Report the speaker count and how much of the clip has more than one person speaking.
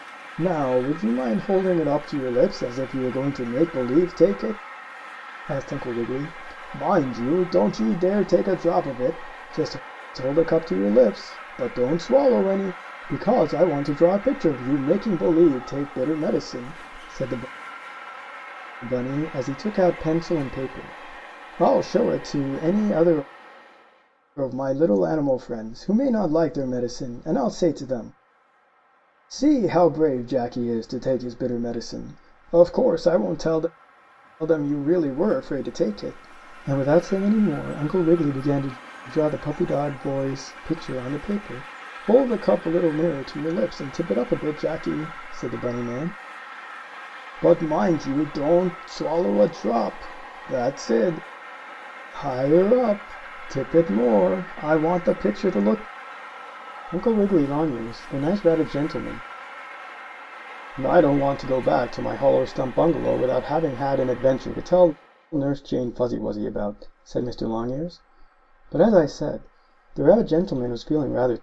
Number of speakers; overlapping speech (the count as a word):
one, no overlap